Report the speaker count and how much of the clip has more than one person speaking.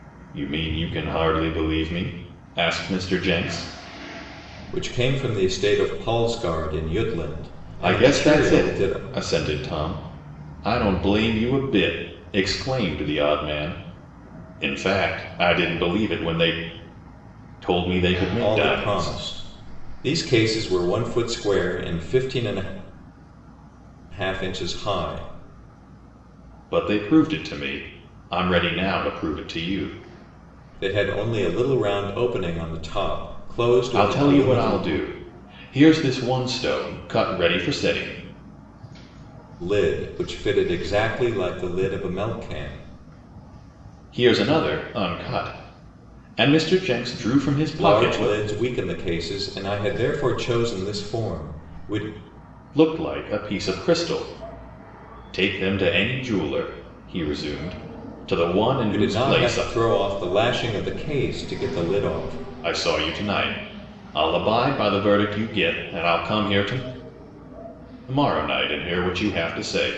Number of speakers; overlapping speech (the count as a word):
two, about 6%